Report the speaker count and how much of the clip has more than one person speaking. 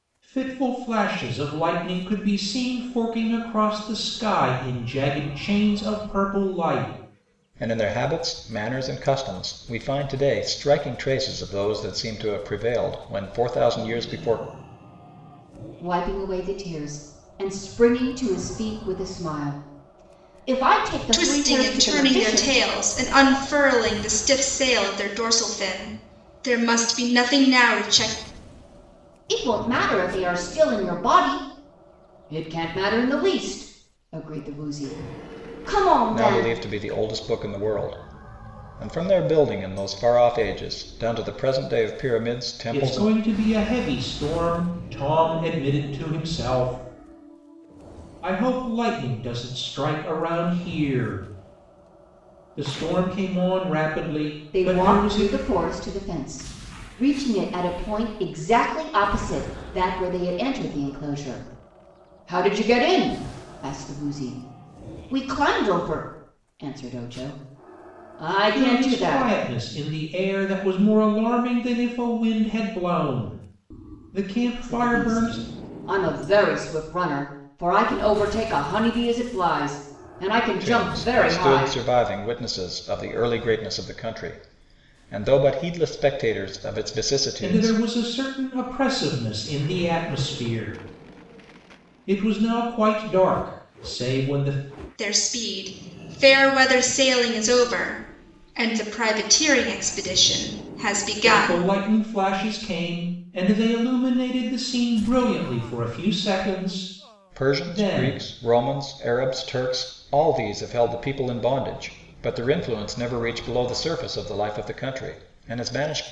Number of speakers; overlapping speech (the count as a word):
four, about 7%